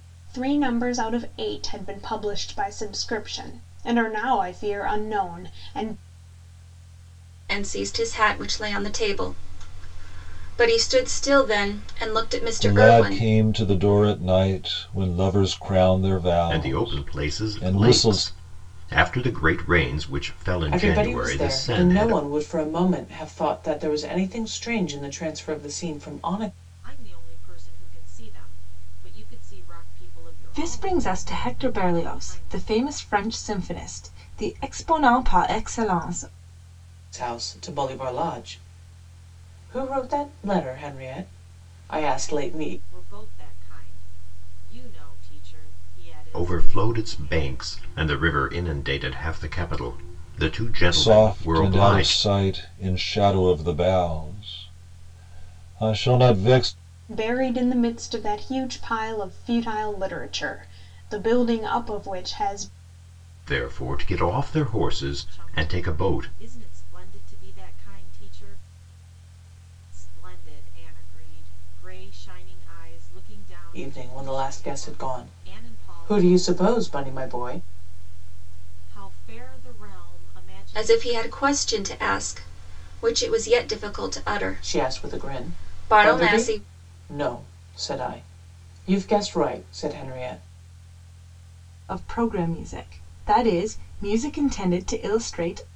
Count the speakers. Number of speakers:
7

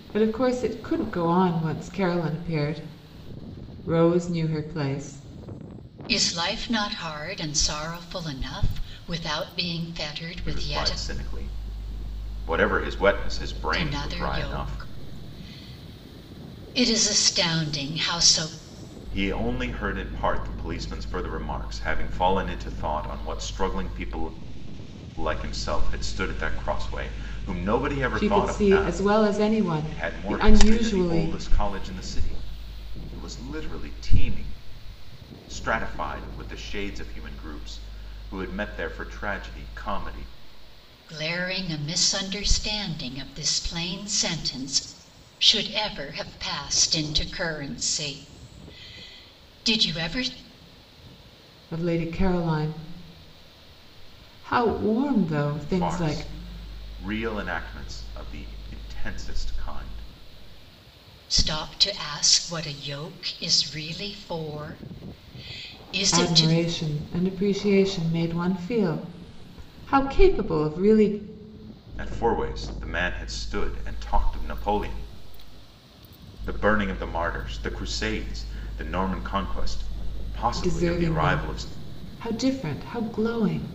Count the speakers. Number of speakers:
3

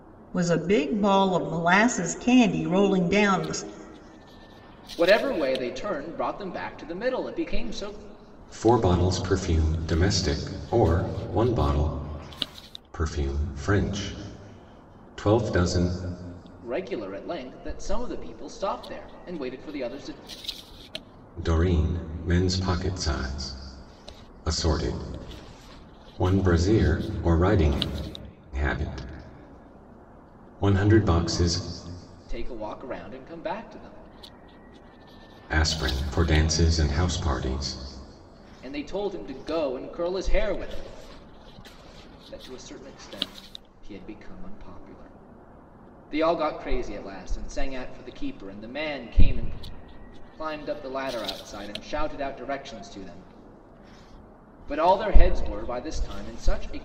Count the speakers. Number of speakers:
3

